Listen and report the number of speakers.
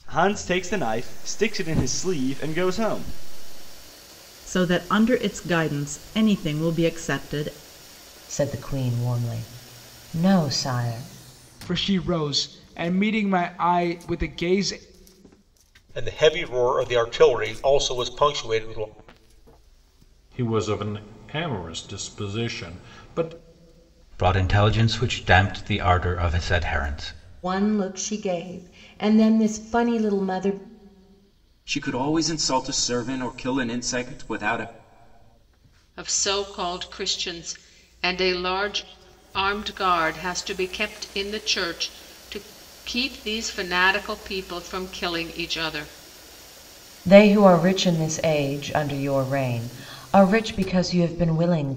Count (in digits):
10